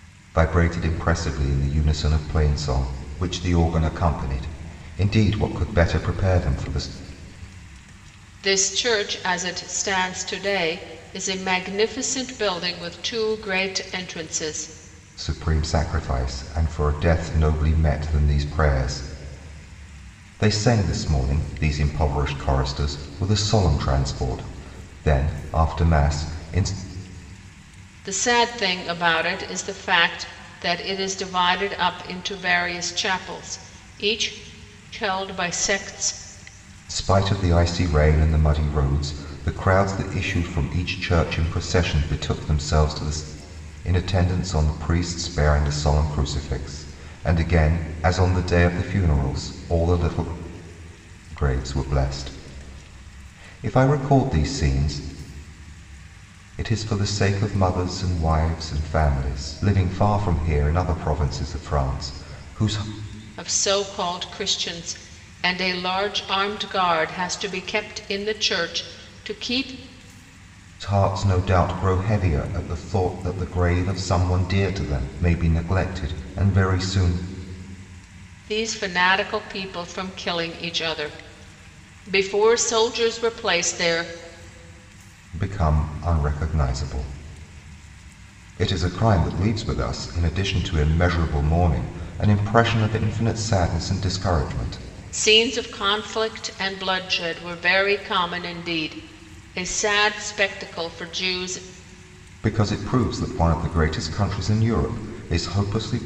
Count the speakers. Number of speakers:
2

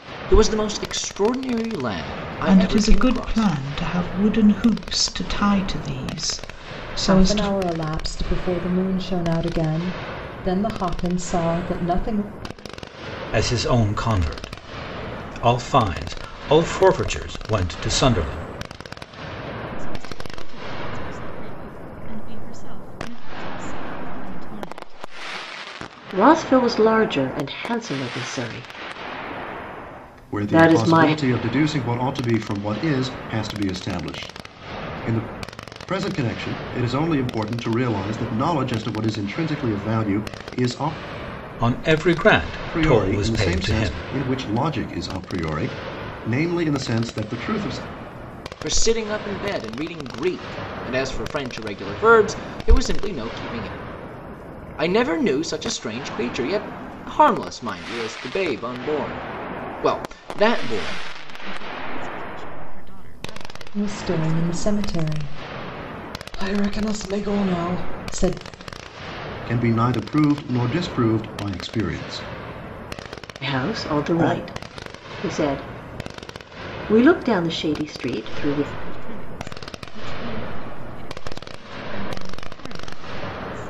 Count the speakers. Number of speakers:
7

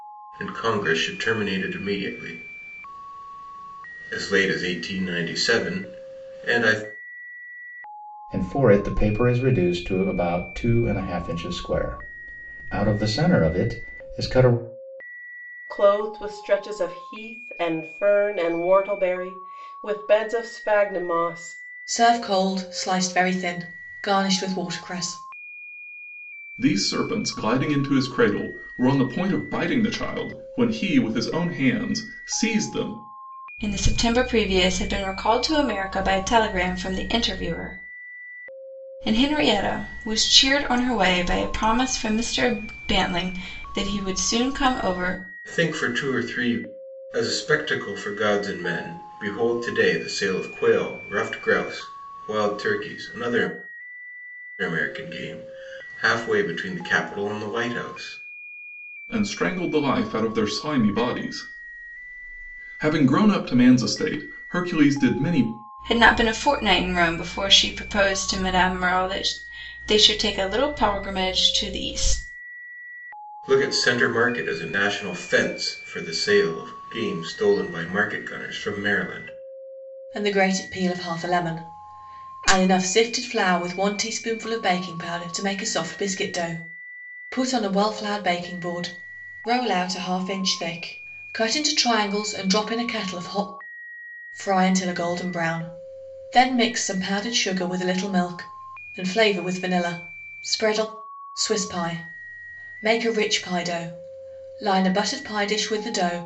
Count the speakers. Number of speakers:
6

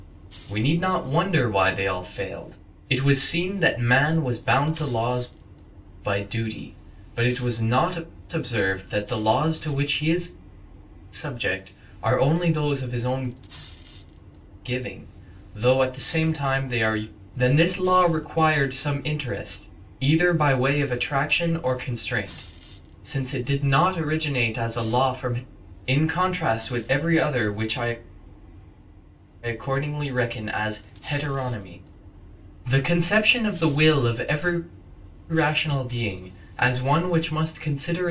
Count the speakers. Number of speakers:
1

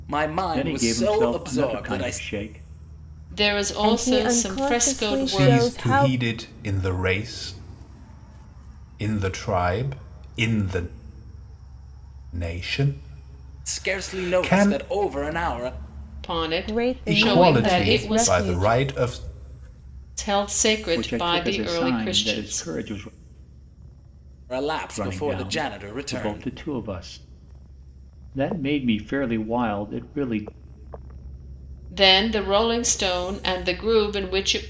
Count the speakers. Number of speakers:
5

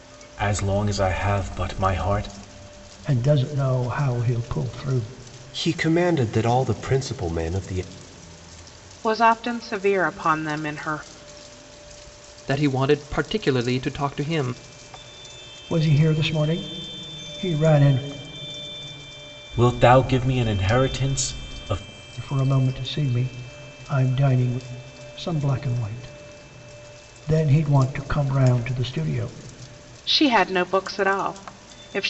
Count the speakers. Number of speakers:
5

